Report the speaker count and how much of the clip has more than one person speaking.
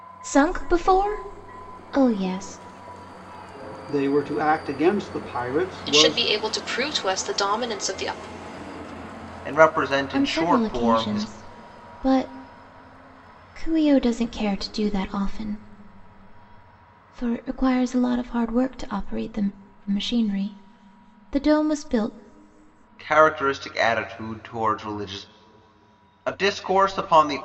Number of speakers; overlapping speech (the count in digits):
4, about 6%